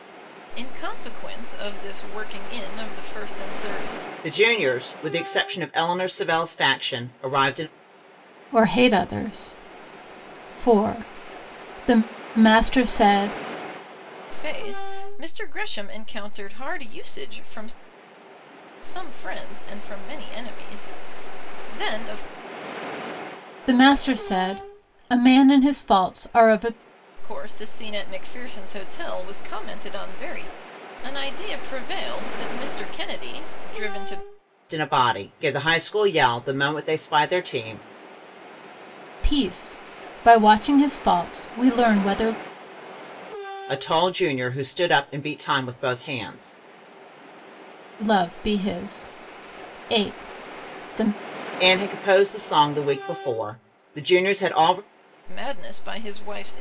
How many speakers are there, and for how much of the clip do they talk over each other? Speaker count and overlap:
3, no overlap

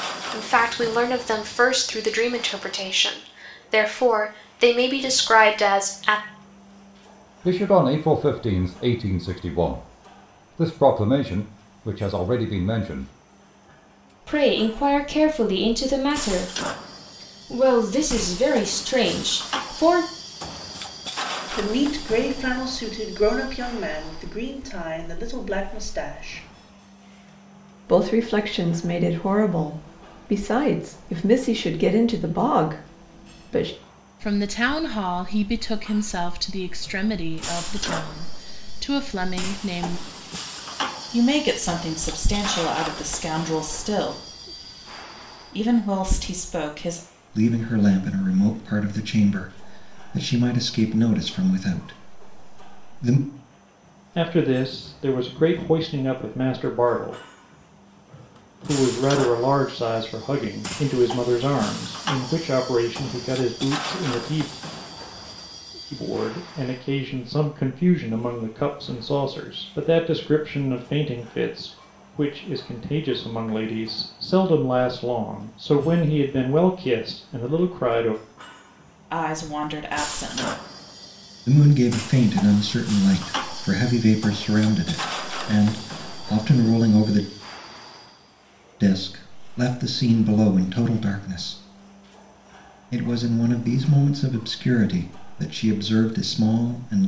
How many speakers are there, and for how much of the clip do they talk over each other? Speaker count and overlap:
9, no overlap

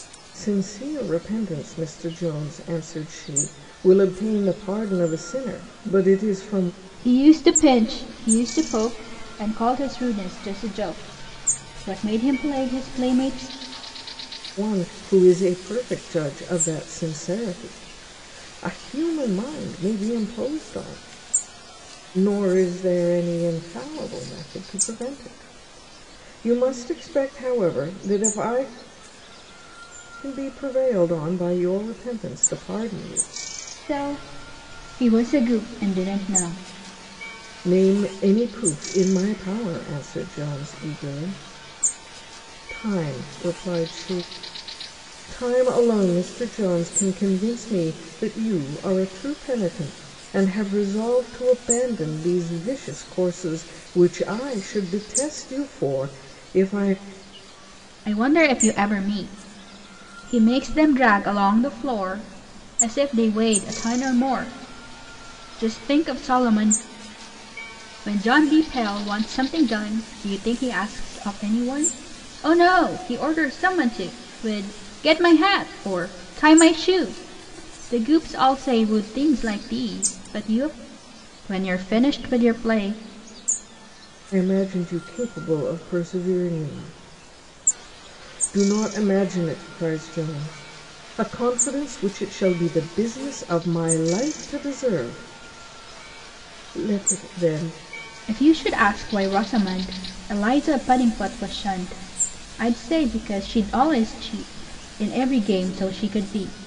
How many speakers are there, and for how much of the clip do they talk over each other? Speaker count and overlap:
2, no overlap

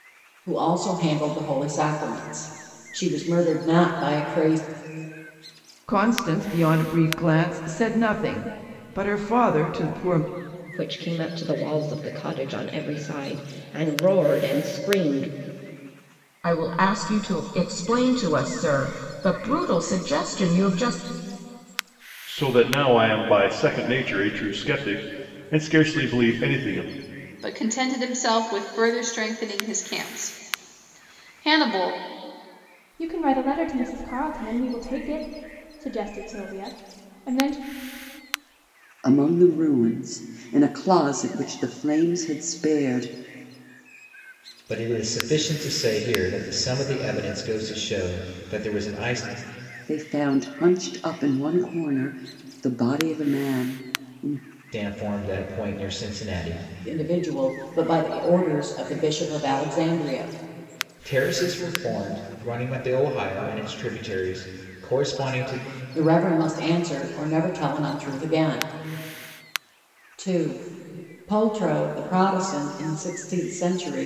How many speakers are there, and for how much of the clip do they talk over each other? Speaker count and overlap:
9, no overlap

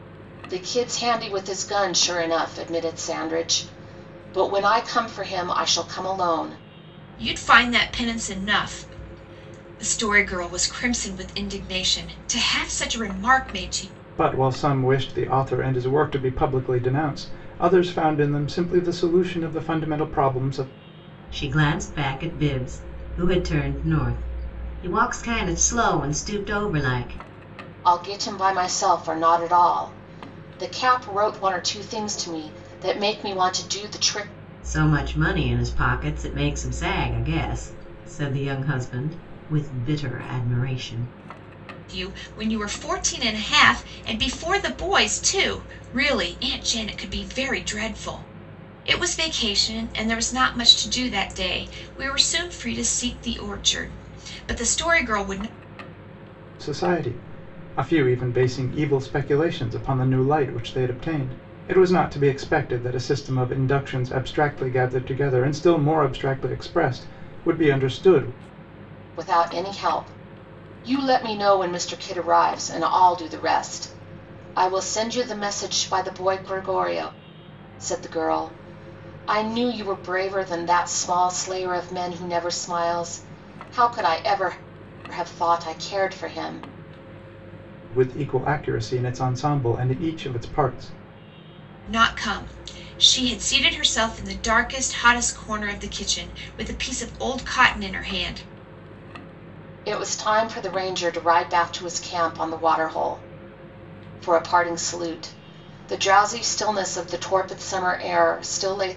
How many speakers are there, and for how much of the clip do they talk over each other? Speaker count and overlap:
4, no overlap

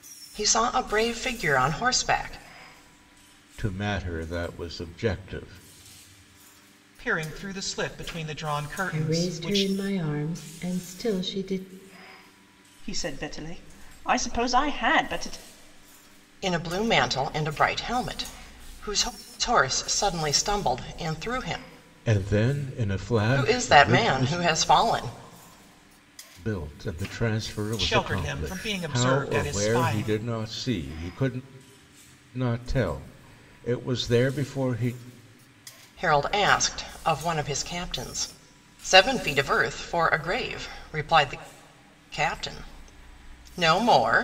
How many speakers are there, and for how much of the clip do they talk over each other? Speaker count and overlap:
5, about 10%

